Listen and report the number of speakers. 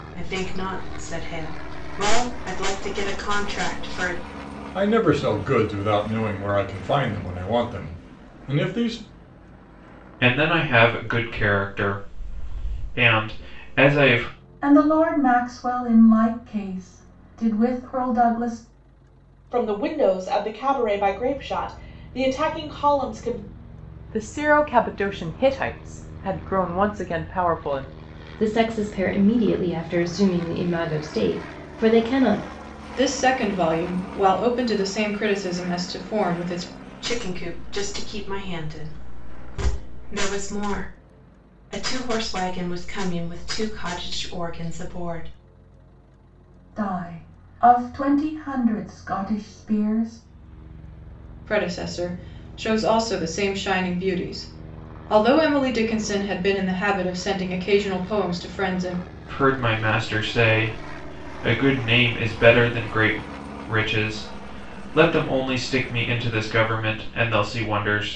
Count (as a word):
eight